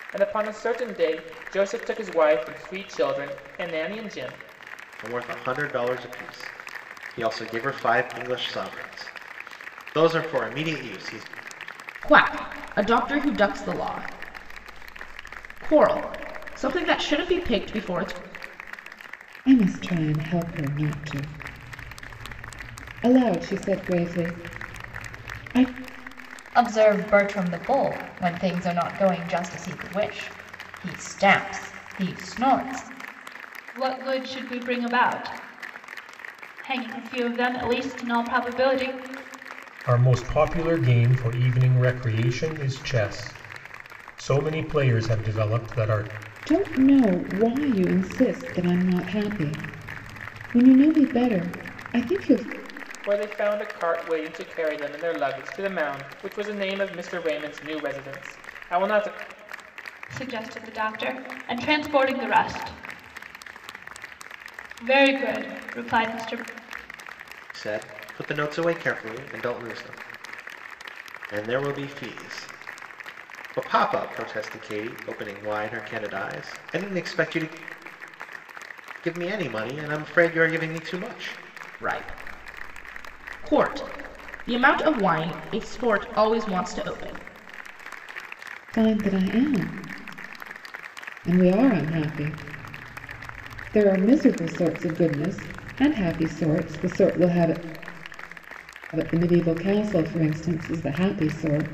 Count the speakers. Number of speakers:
7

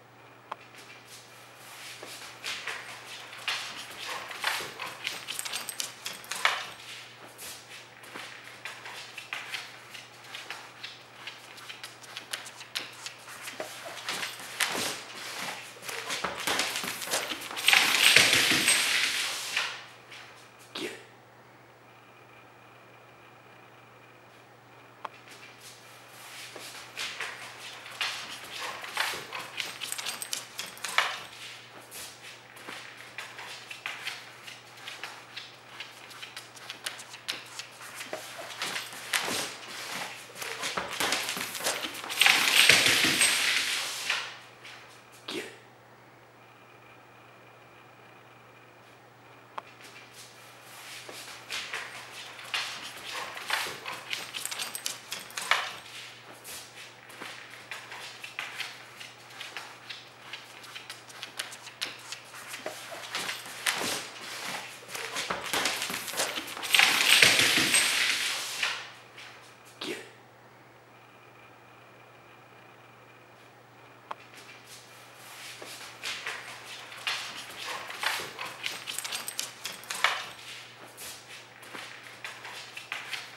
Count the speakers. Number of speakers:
0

